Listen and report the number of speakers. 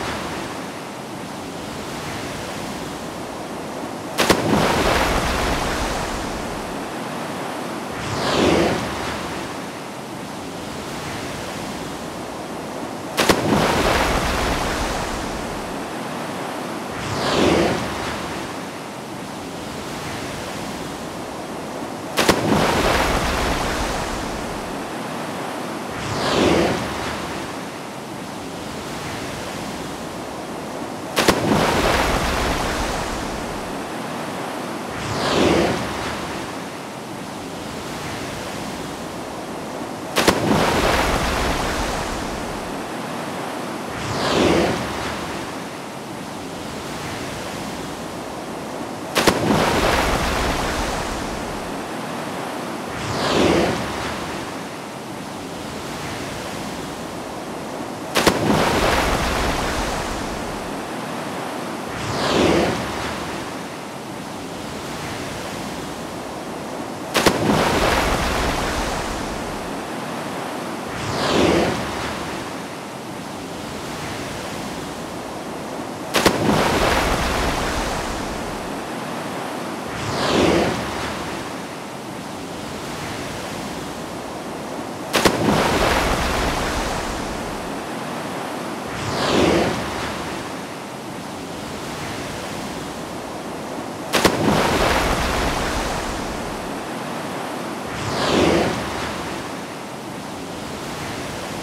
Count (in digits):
0